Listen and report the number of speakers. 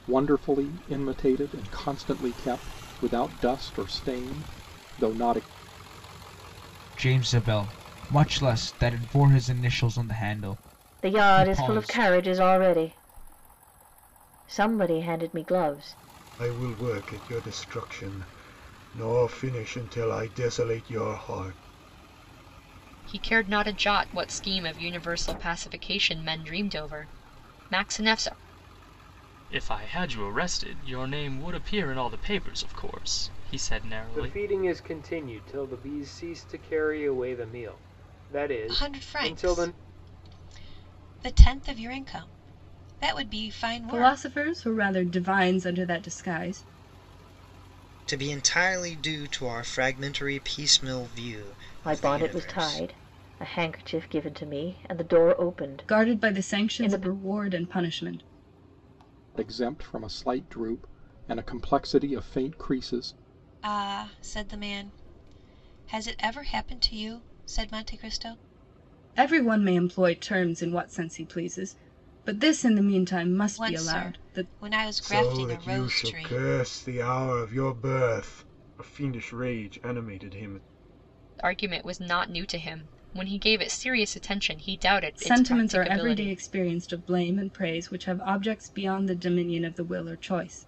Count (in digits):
10